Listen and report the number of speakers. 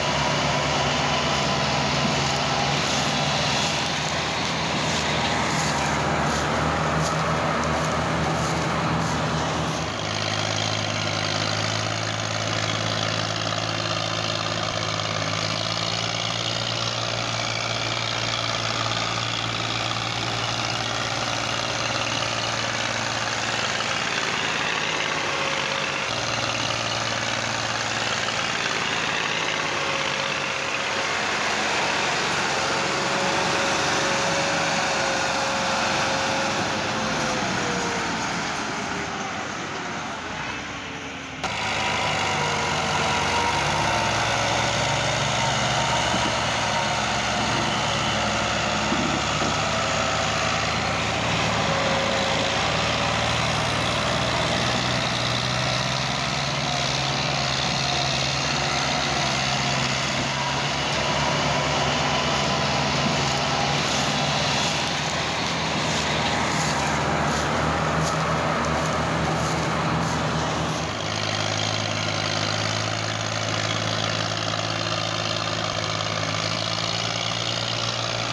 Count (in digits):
0